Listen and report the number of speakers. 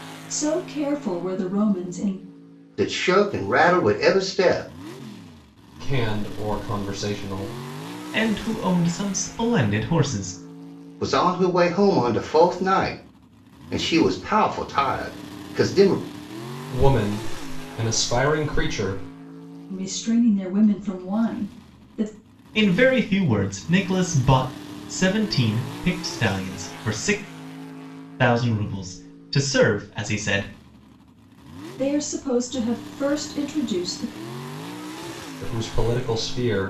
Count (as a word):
four